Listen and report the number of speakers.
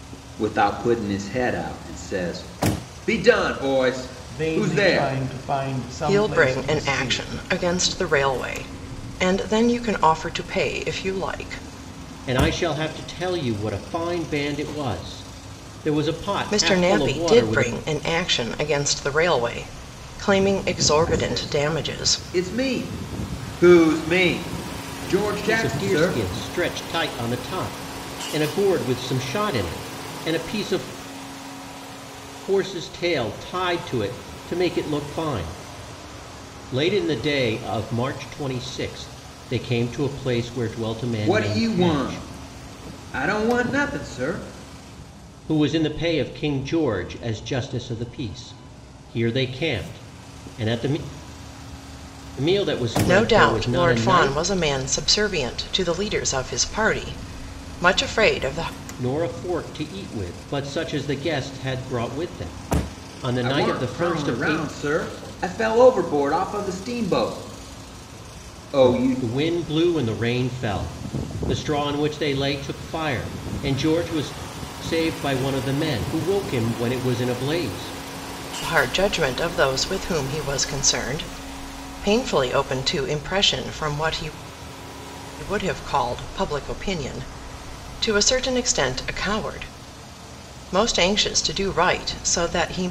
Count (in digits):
4